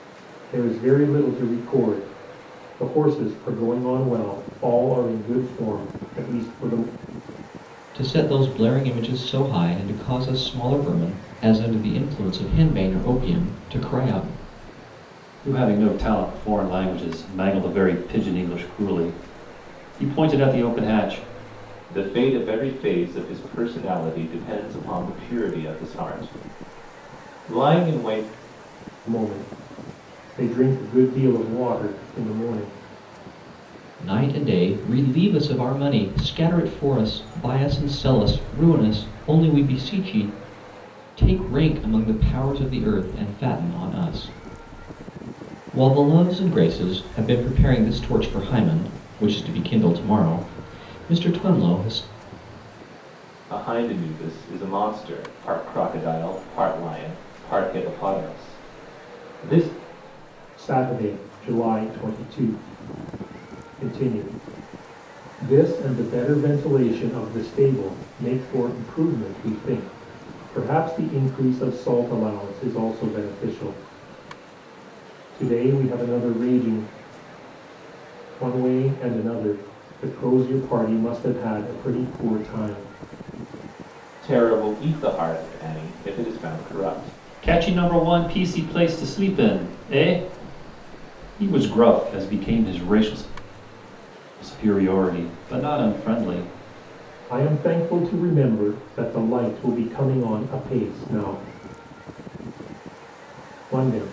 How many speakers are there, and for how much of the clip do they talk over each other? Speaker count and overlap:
four, no overlap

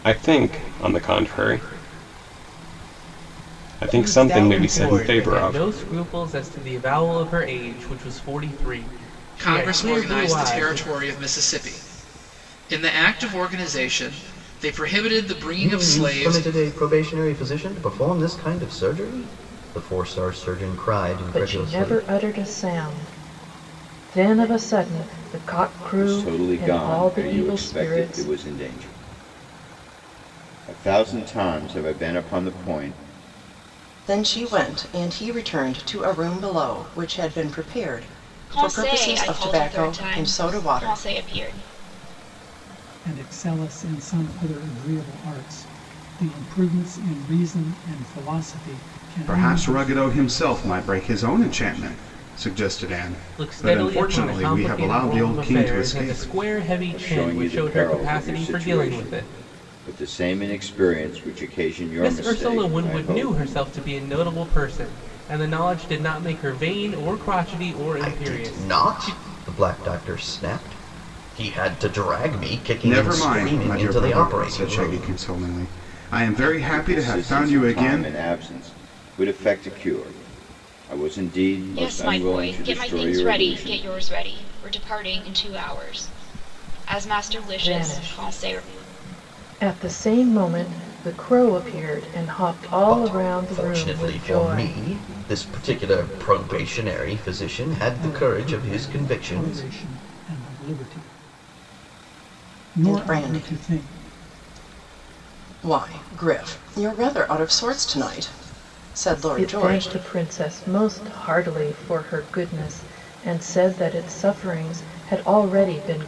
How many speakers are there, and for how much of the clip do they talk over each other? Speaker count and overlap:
ten, about 27%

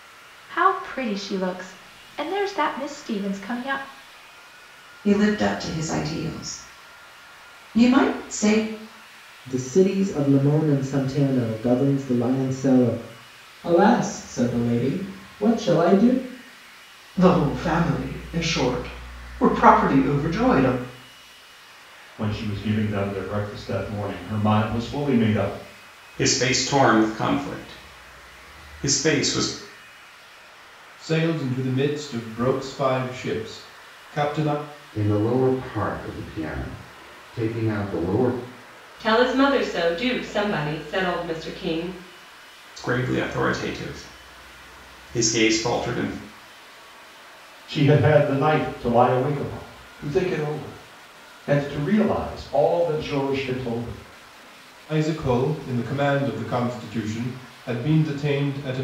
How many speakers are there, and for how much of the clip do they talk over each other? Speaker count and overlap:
ten, no overlap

